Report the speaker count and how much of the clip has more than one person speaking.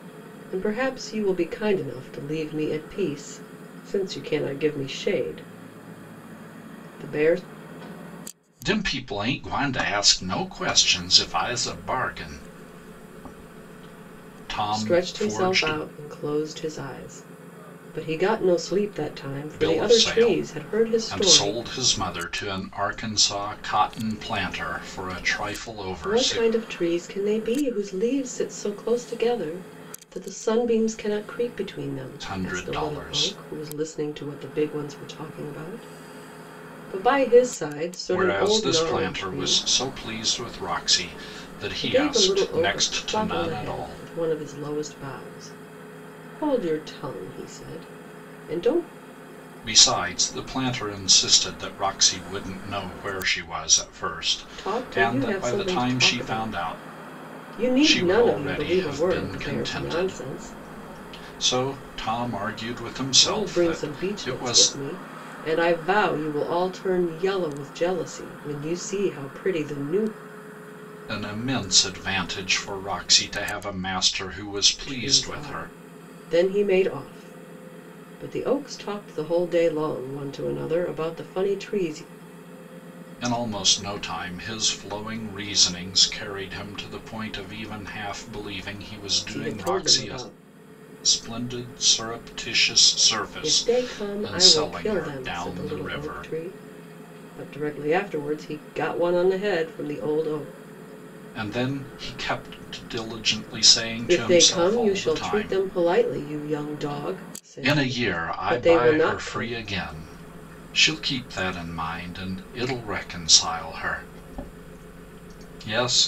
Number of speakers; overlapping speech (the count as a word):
two, about 20%